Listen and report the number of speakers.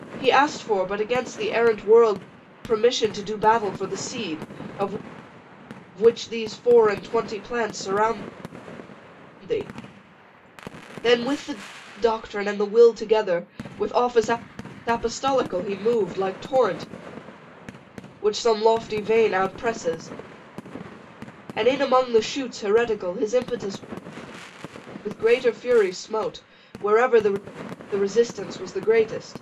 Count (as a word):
one